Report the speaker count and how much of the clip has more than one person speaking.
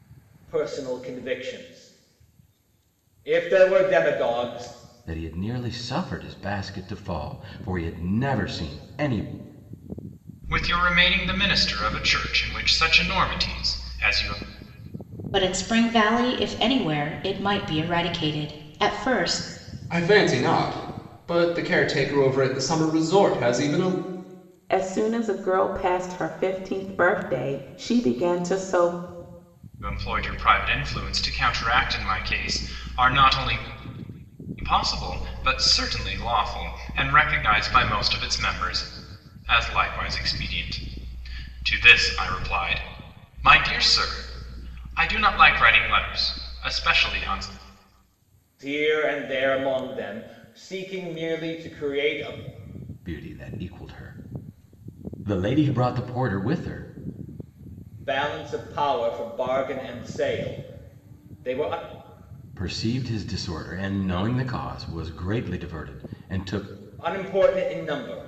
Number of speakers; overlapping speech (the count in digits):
6, no overlap